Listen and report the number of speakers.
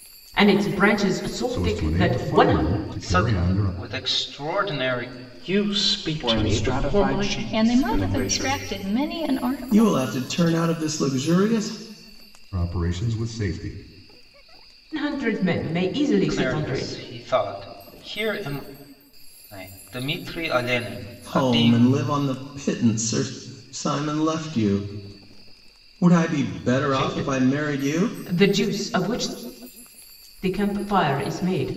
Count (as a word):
seven